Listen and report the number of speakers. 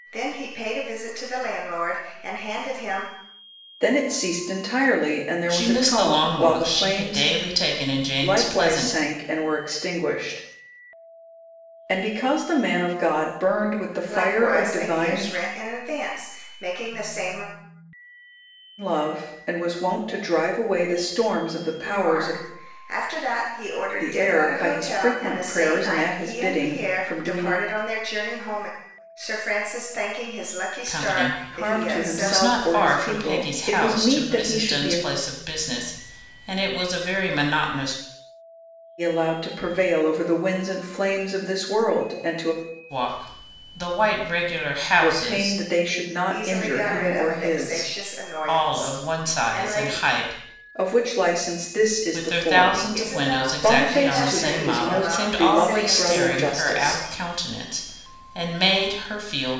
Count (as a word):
three